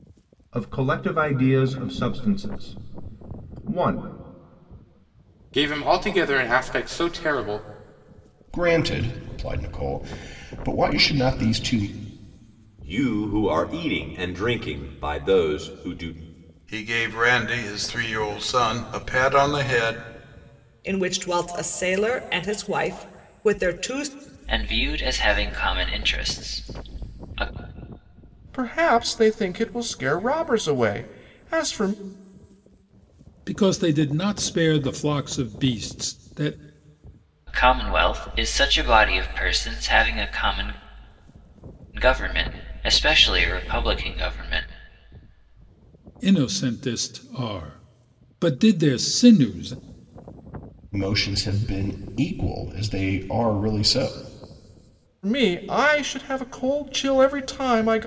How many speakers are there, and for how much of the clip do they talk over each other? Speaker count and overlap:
9, no overlap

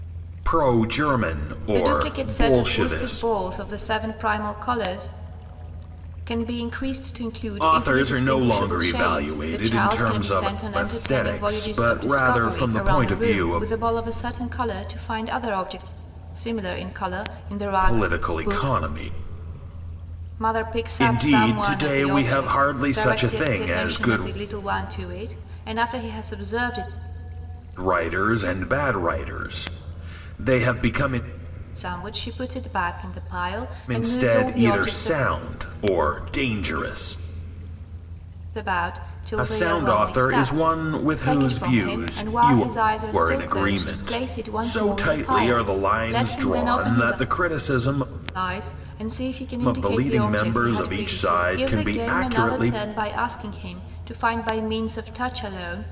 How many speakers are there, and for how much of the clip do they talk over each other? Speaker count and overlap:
2, about 41%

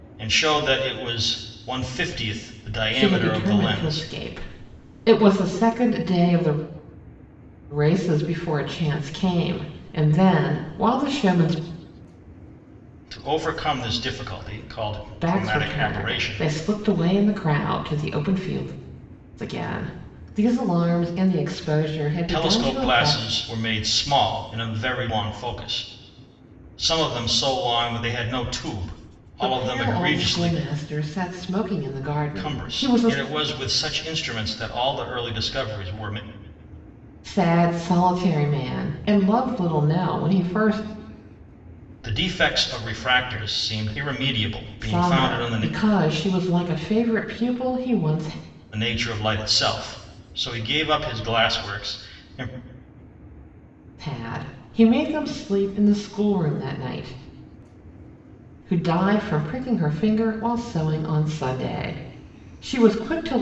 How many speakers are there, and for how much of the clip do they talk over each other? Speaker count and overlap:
2, about 10%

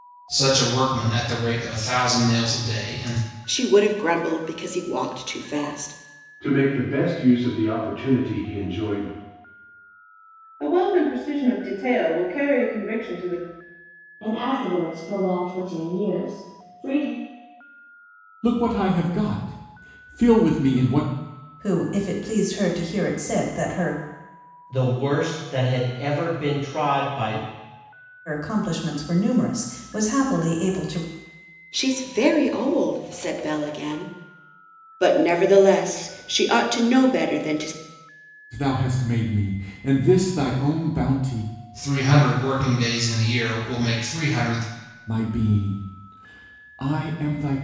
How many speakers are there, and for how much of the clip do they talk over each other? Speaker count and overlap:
8, no overlap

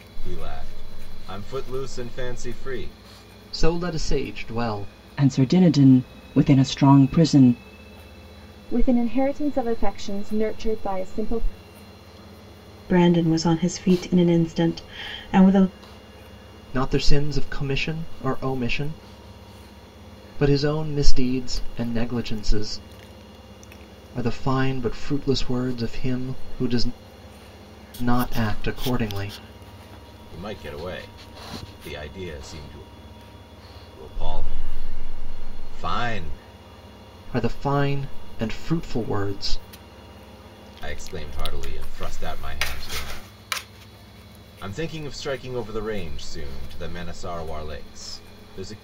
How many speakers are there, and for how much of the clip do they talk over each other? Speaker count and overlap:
5, no overlap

